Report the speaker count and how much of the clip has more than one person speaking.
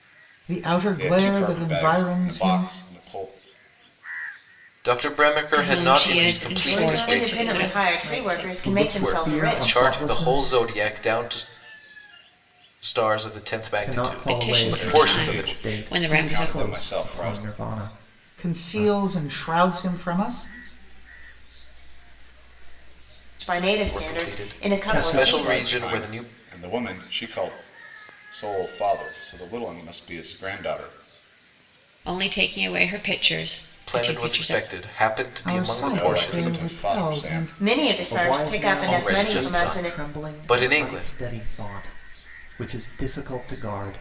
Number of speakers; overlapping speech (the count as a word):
seven, about 49%